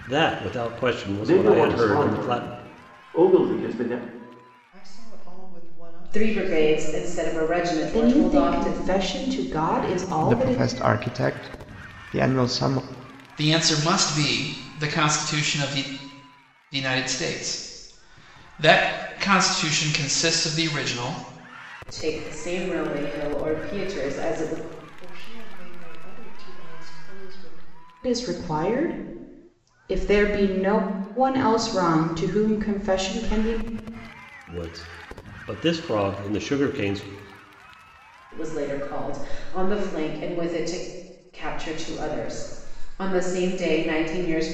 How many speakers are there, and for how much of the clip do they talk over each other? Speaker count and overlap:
7, about 8%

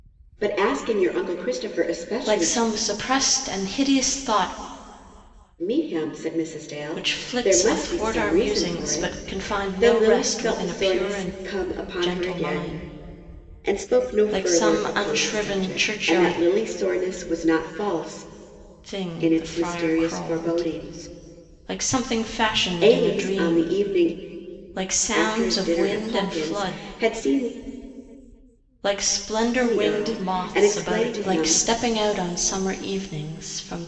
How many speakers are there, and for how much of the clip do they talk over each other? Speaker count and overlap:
2, about 44%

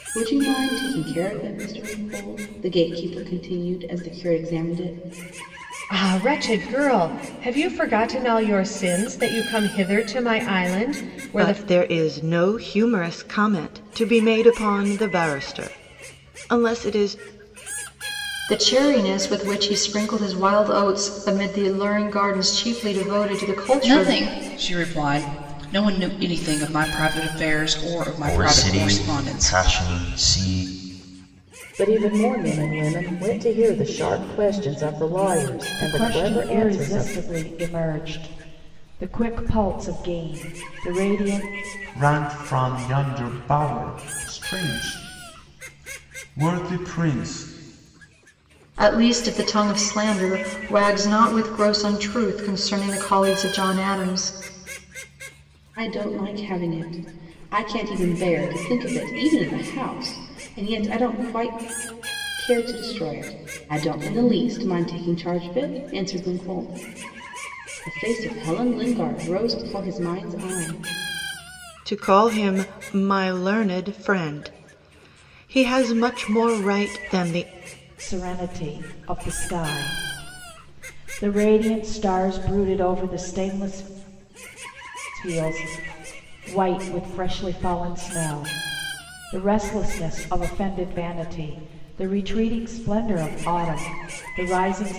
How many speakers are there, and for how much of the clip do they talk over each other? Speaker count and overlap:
9, about 4%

